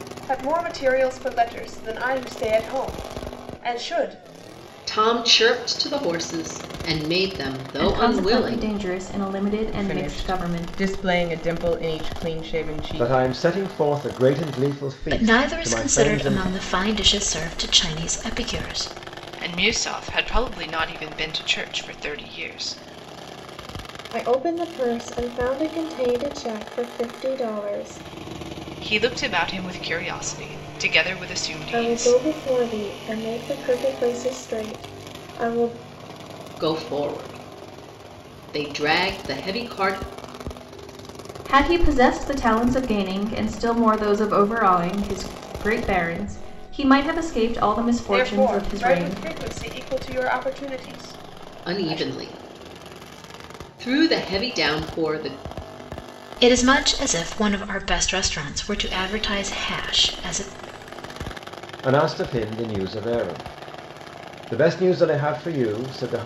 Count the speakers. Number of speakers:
8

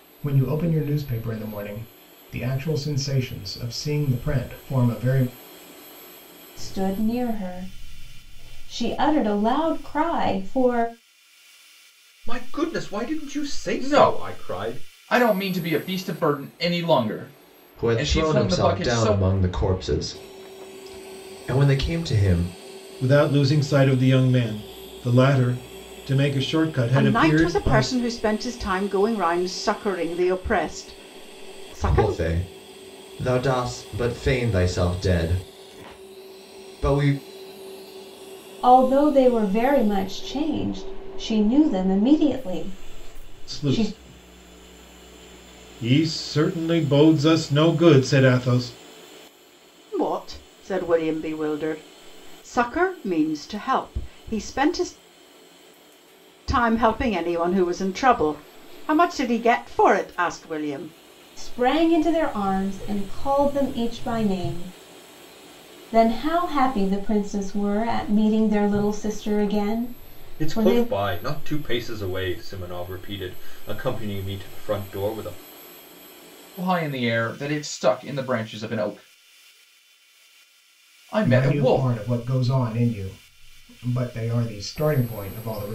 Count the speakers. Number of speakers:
7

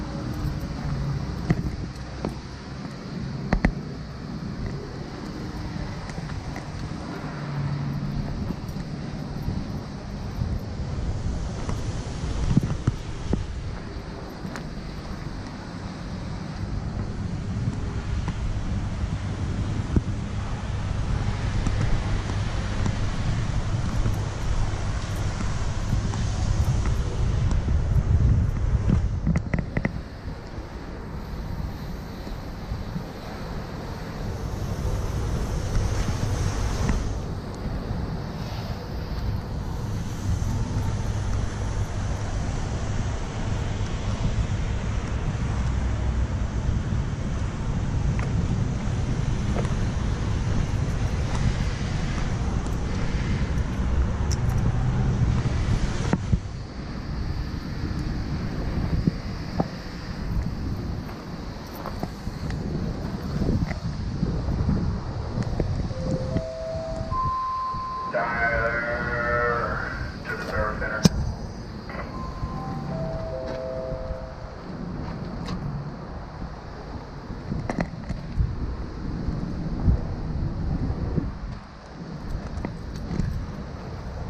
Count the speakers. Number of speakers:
0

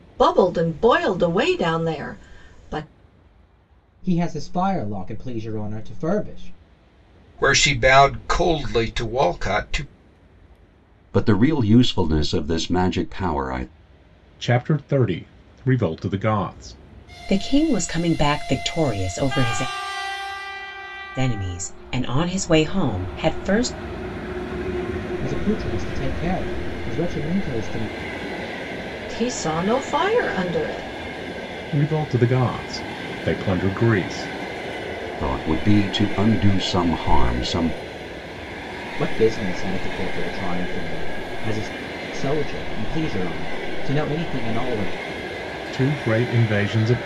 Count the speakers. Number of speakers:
6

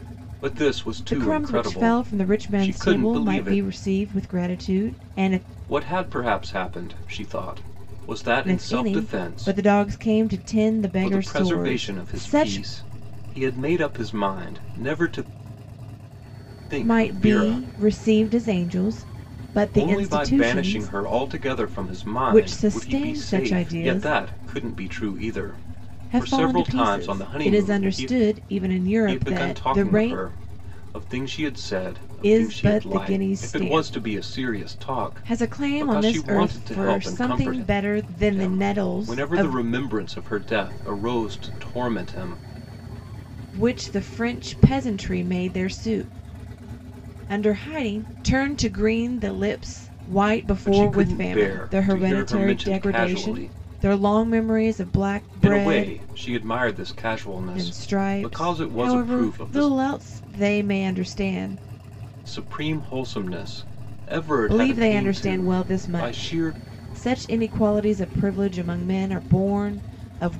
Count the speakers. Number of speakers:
2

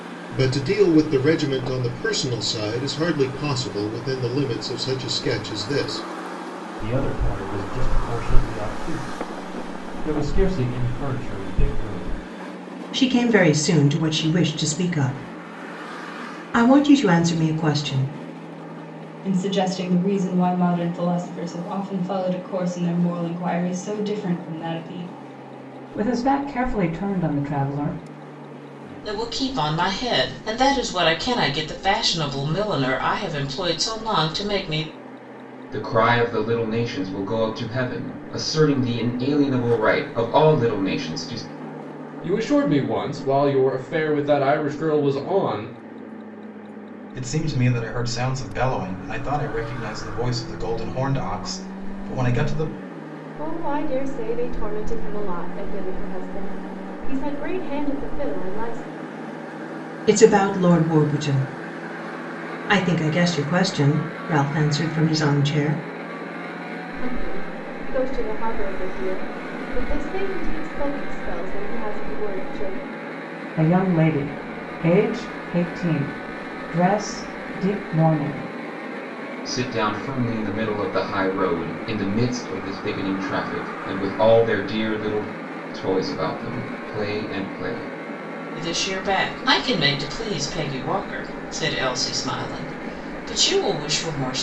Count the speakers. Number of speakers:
10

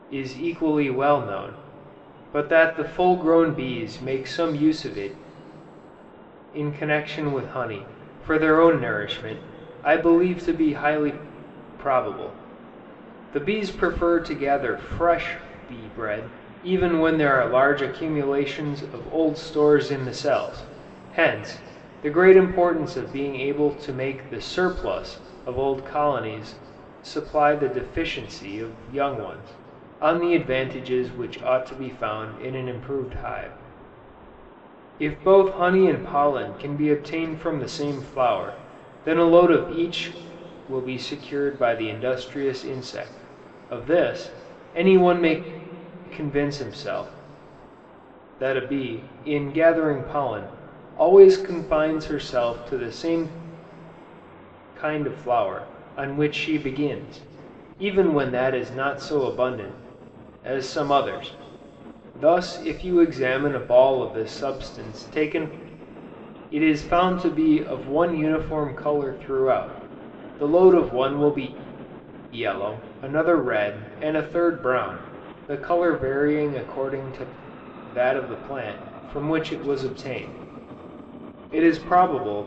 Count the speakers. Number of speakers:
1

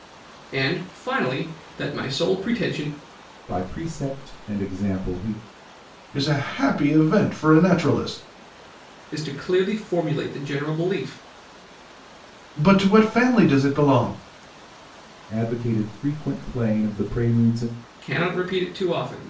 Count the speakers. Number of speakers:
3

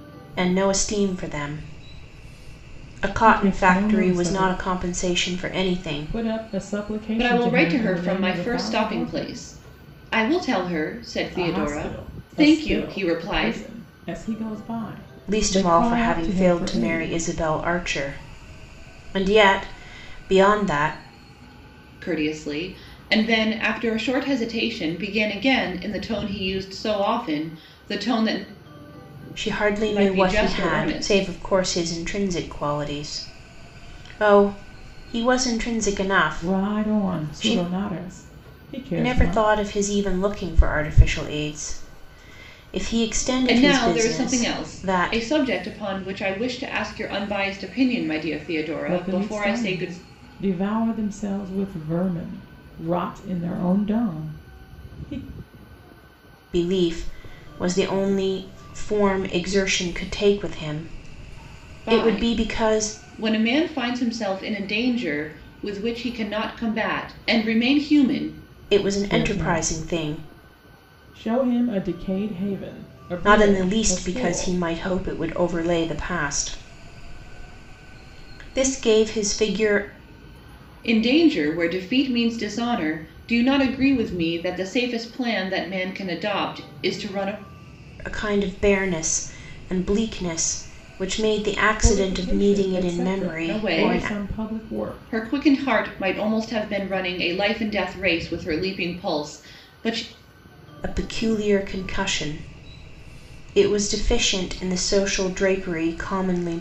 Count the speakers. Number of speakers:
3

